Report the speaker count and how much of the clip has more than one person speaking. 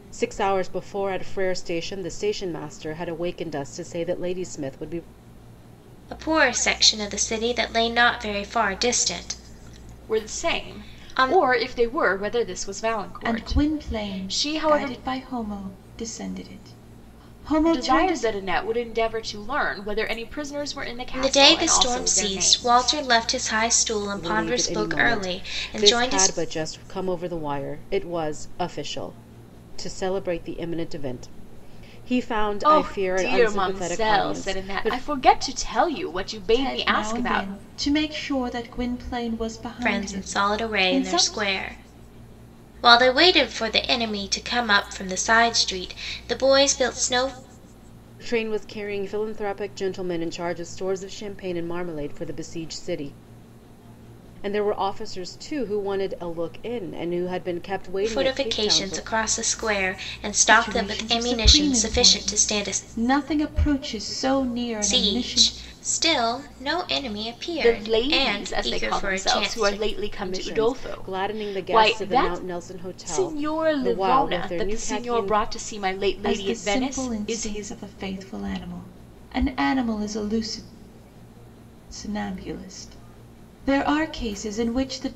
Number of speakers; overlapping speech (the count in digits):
4, about 30%